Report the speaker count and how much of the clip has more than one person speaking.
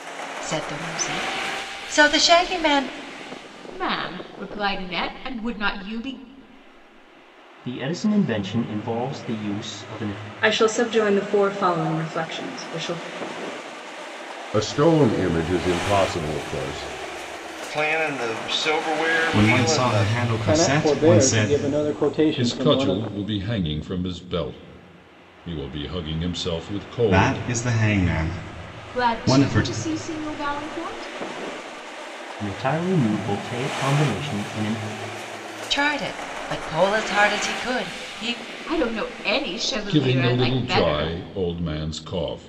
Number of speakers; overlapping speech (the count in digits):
9, about 13%